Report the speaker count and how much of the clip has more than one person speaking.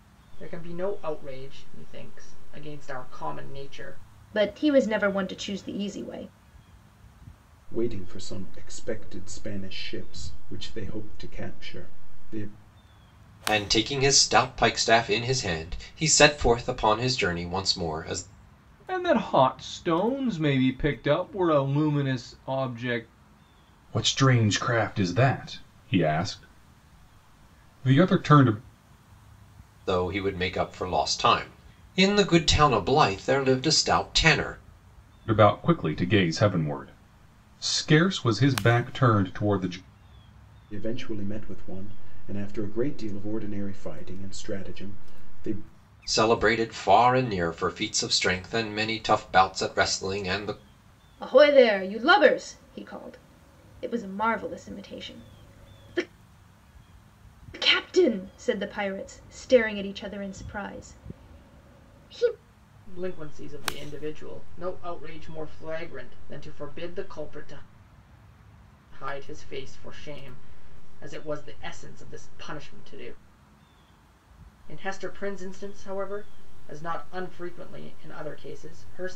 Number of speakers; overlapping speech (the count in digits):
6, no overlap